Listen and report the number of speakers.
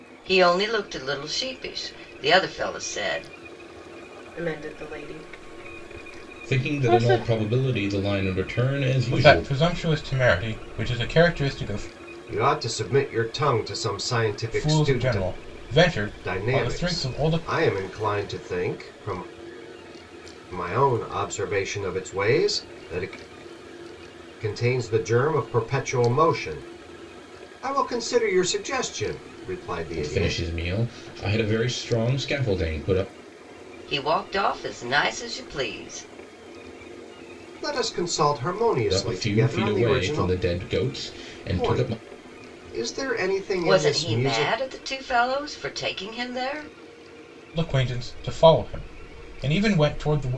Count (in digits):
5